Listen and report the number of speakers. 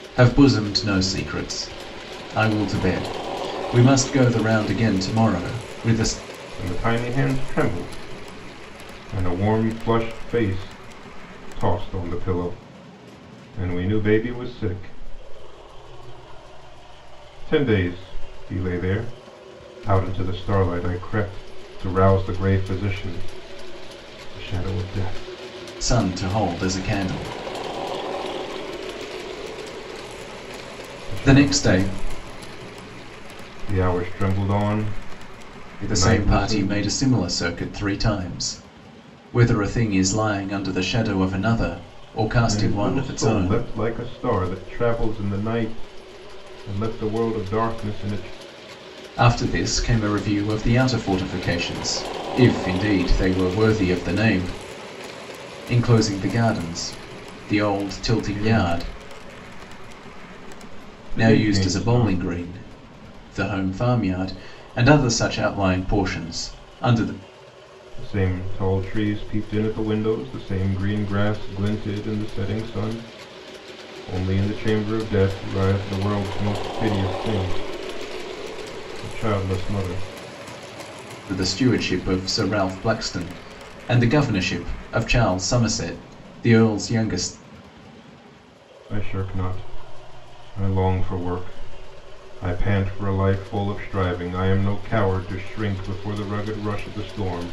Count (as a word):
two